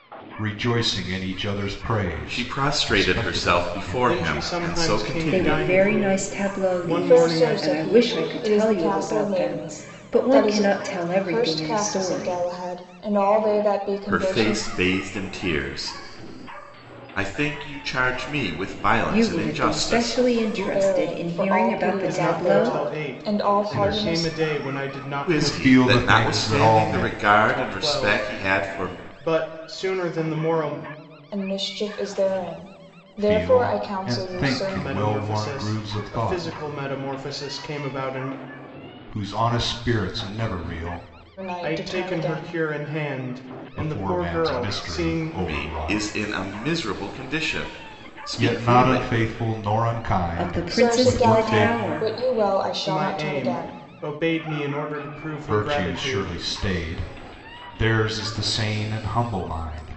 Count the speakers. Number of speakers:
five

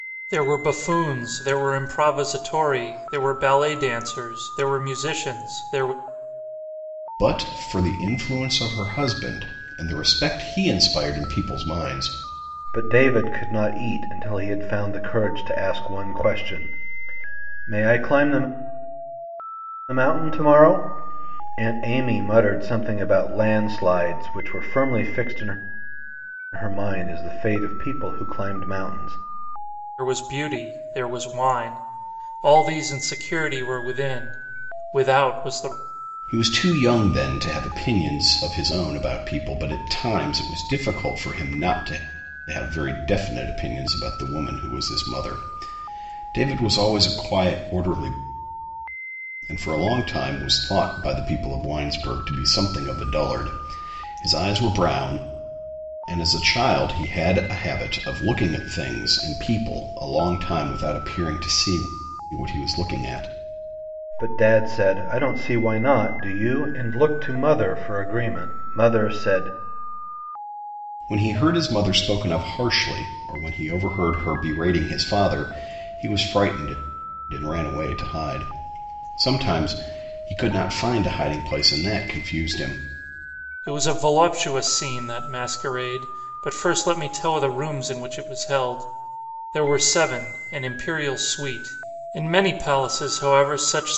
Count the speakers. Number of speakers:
three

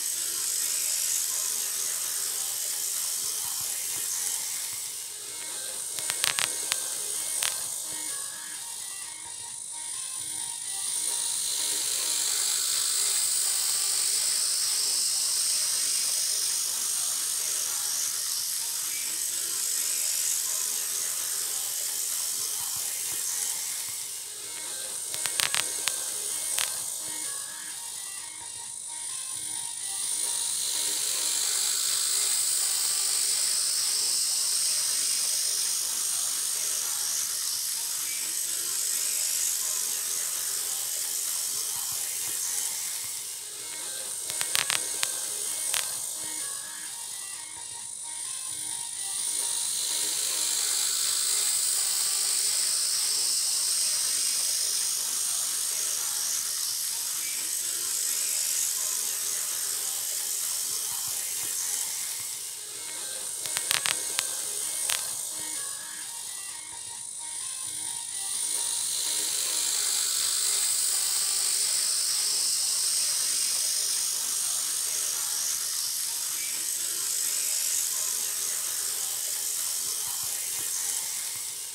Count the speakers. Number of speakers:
zero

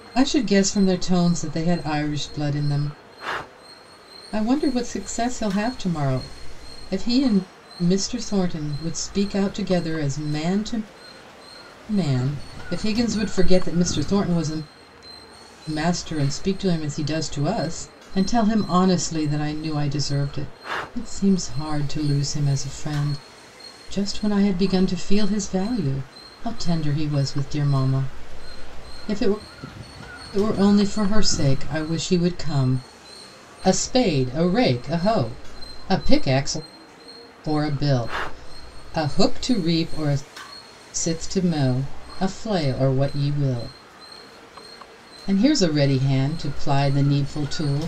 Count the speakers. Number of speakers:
one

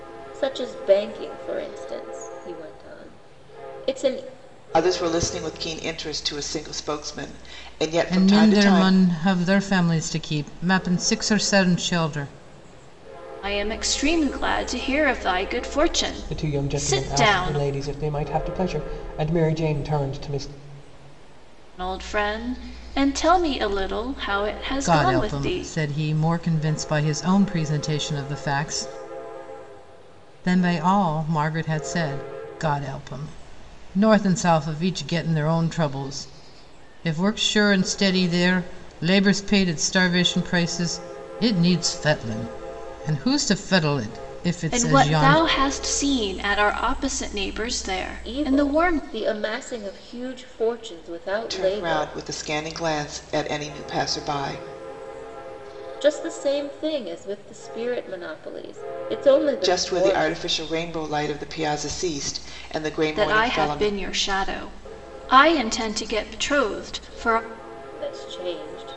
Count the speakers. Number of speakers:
five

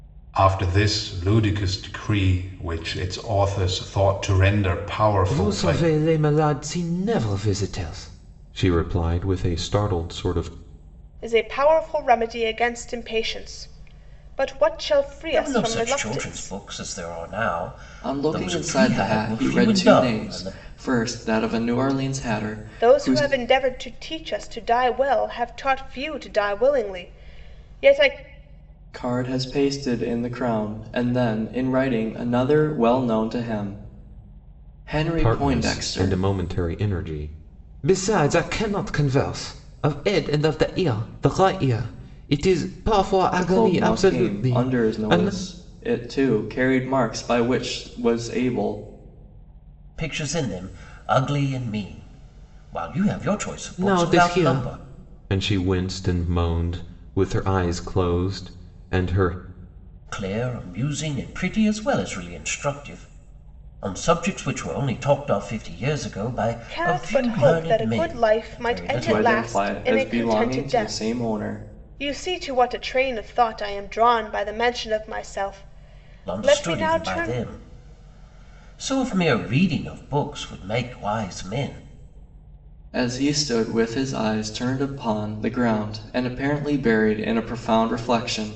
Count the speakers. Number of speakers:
five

